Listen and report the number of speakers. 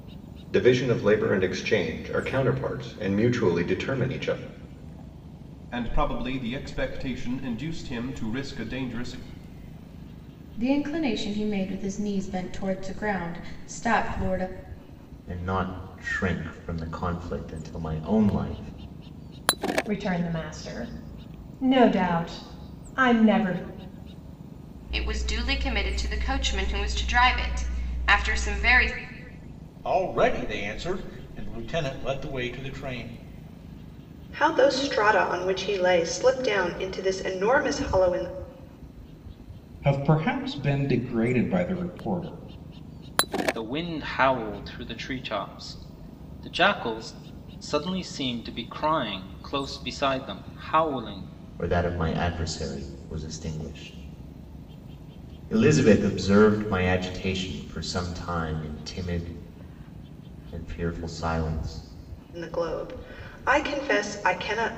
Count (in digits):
10